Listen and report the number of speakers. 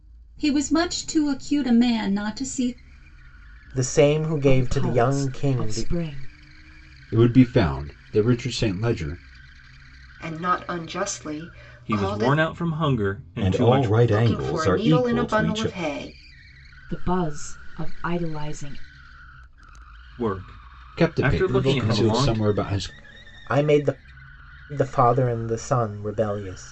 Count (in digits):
7